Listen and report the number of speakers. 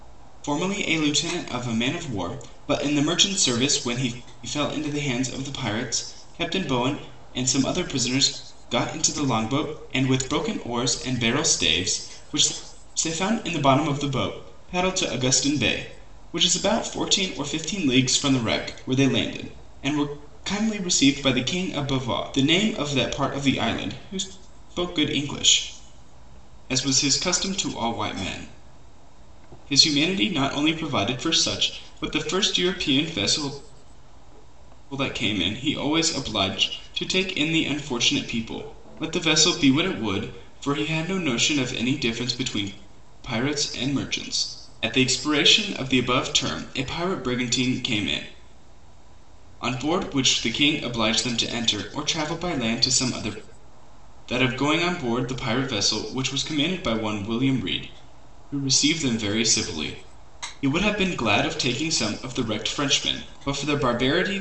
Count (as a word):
one